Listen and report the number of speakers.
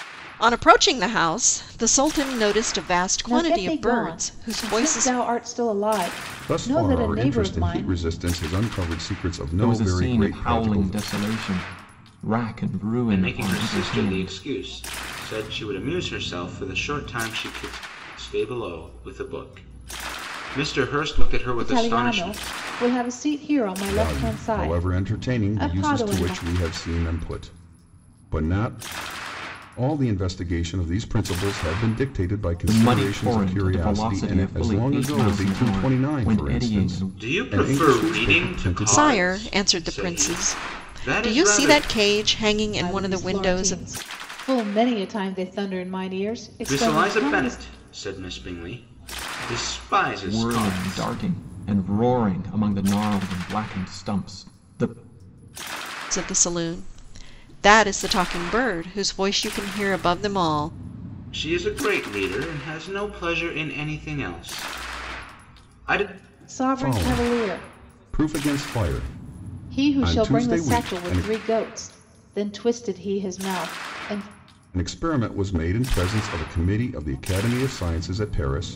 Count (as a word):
five